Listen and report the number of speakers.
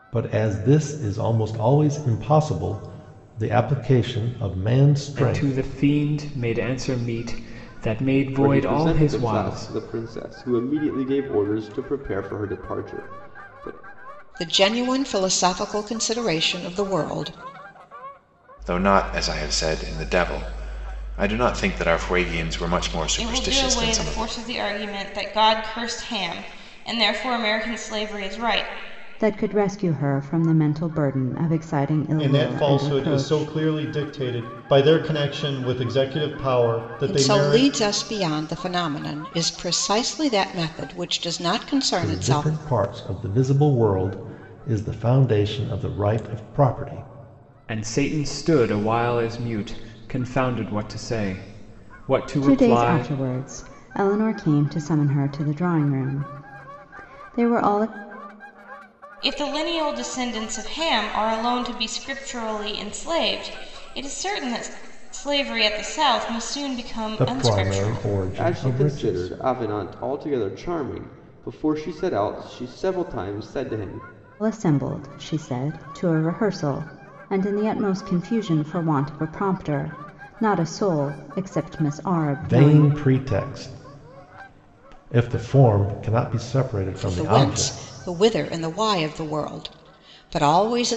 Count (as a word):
eight